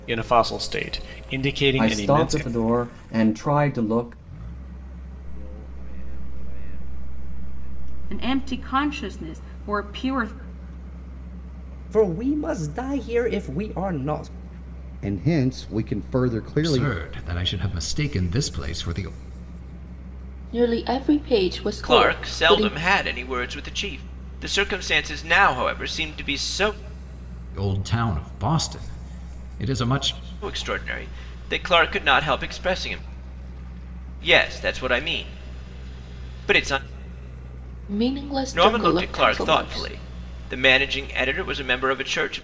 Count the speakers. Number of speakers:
9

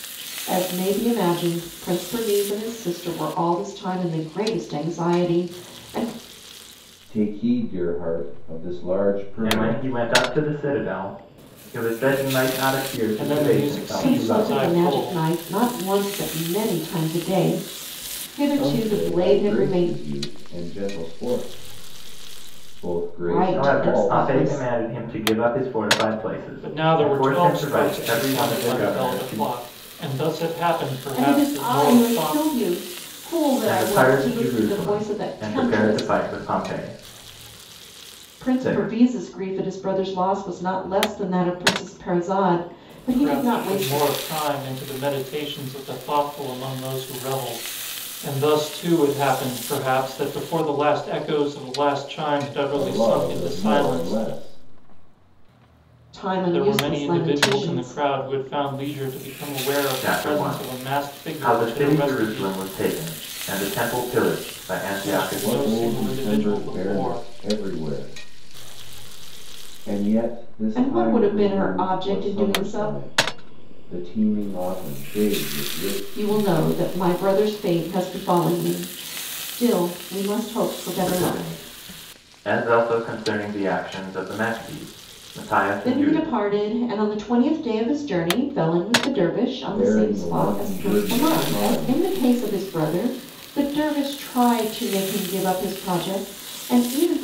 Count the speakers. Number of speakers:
4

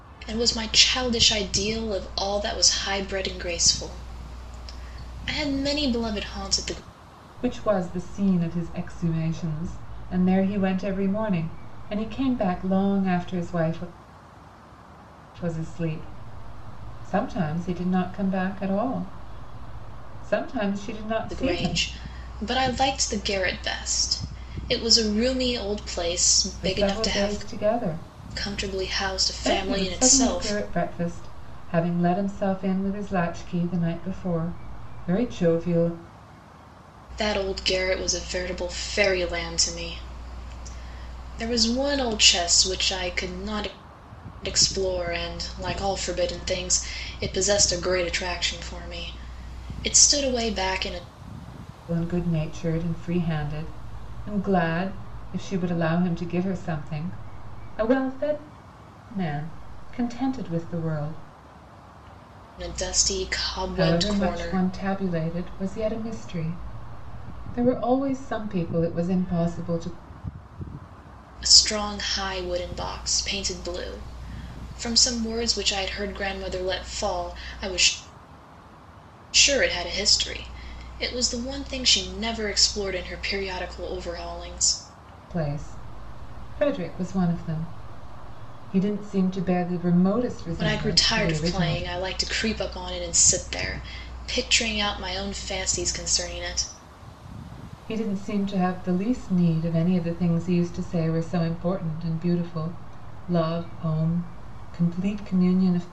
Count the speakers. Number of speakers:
2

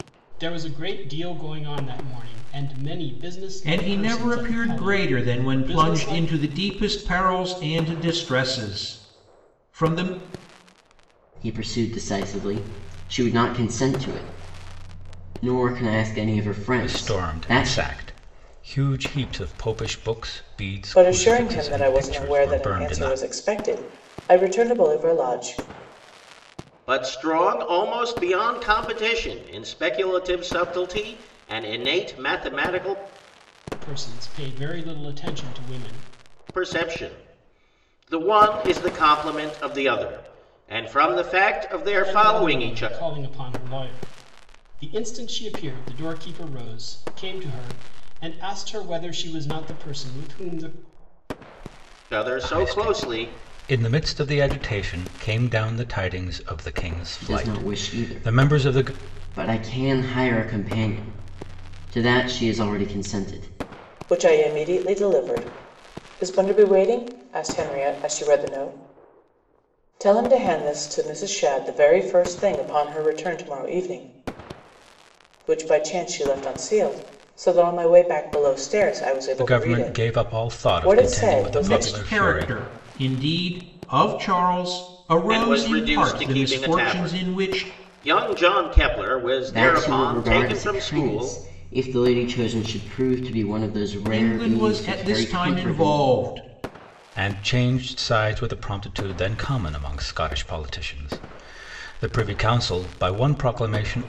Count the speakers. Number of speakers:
6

